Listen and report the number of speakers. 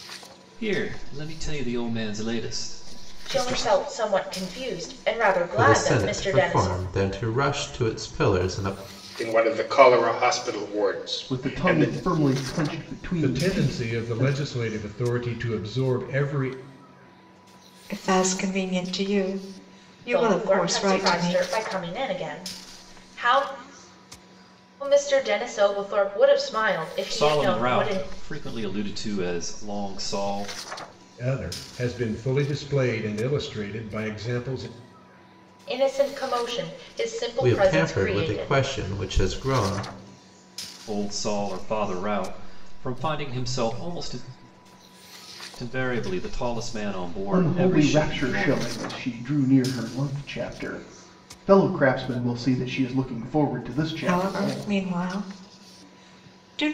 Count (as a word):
seven